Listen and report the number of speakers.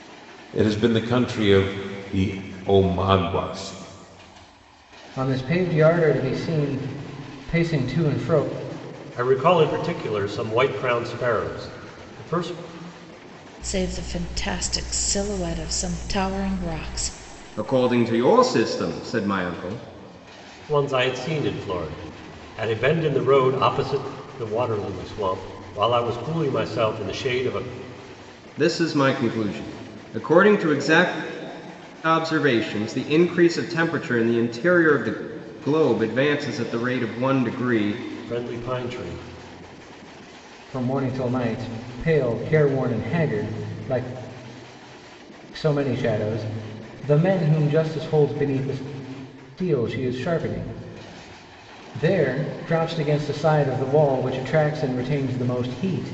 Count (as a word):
five